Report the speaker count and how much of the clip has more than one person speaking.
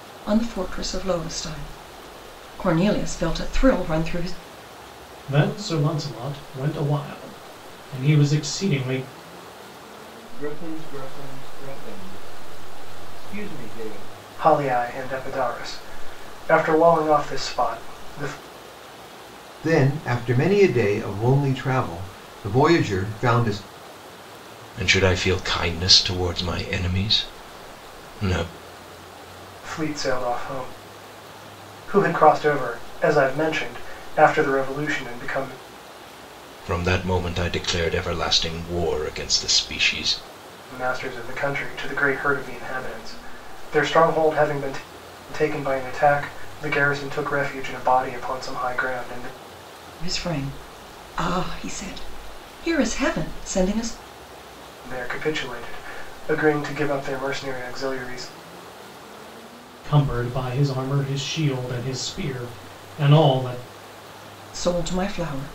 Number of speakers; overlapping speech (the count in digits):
6, no overlap